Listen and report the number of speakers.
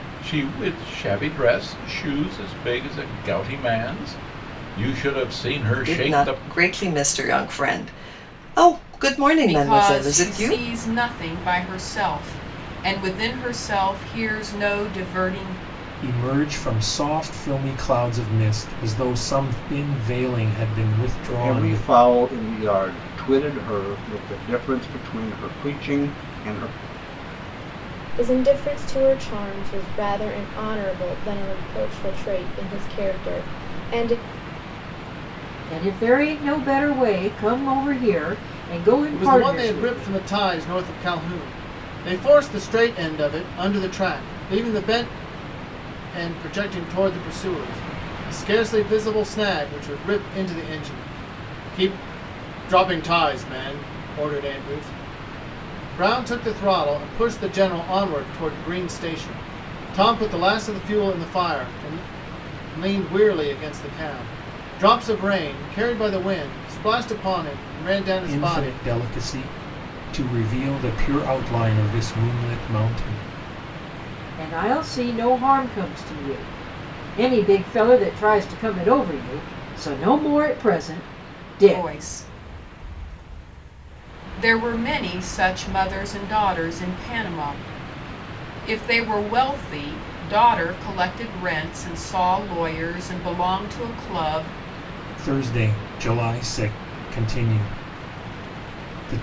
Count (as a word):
eight